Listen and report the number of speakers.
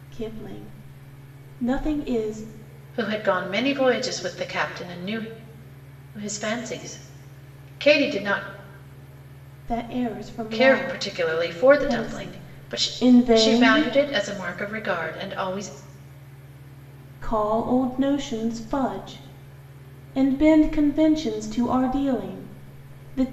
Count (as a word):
two